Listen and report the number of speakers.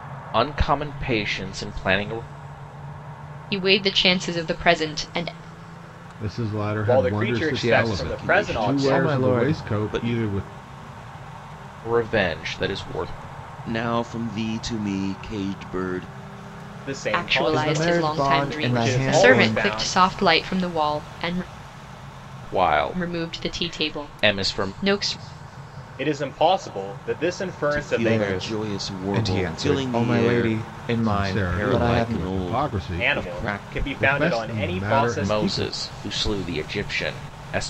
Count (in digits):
6